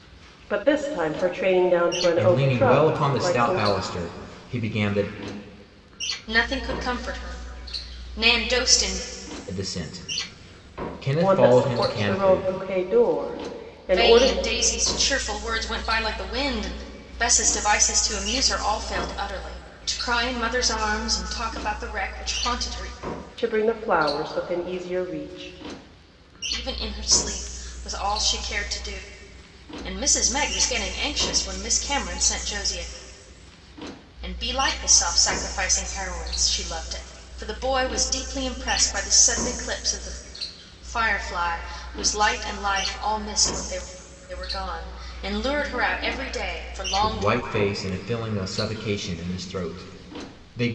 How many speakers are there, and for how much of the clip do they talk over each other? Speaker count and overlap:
3, about 7%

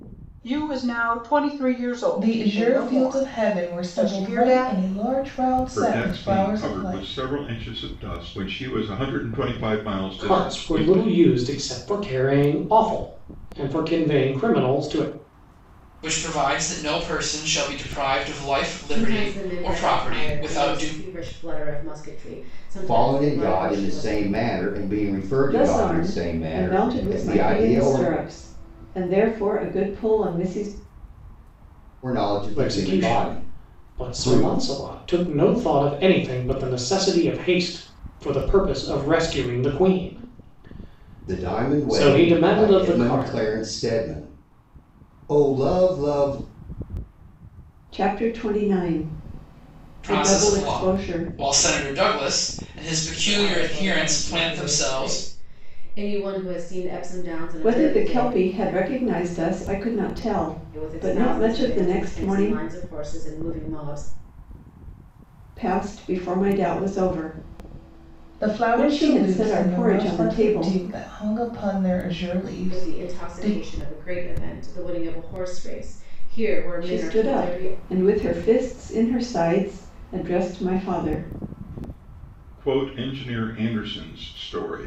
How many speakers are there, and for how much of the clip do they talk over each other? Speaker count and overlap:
8, about 31%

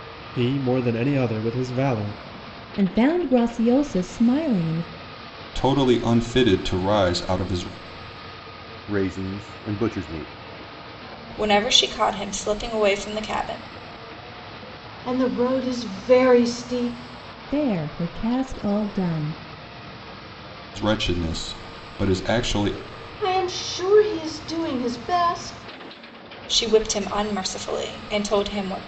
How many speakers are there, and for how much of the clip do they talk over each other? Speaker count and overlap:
6, no overlap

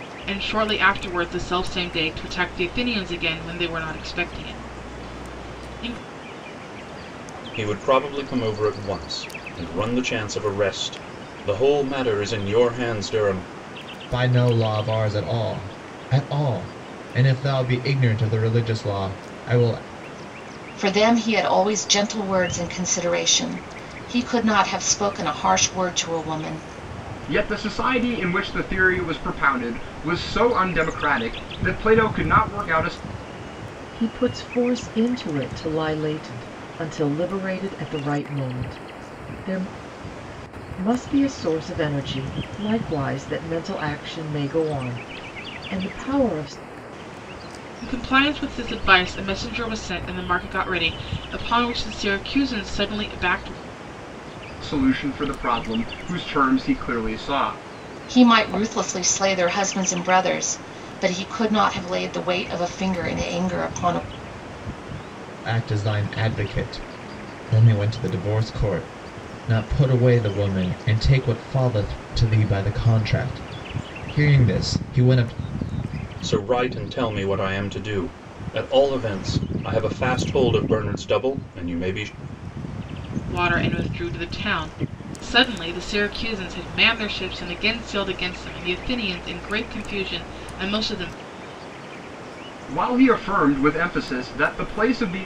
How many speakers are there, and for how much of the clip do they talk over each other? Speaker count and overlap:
6, no overlap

